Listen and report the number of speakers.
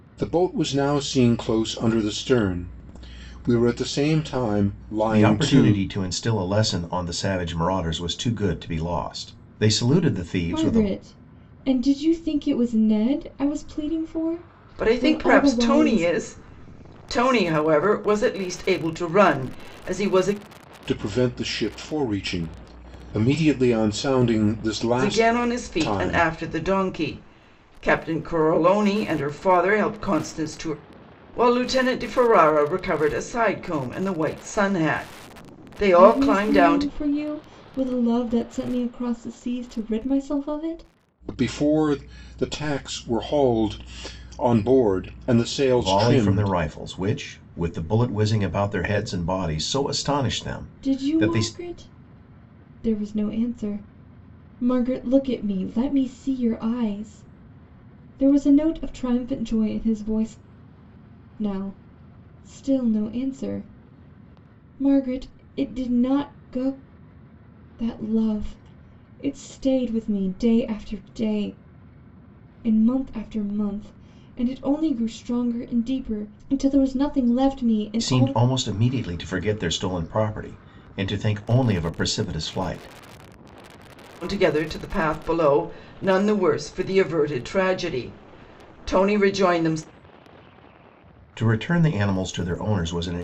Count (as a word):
four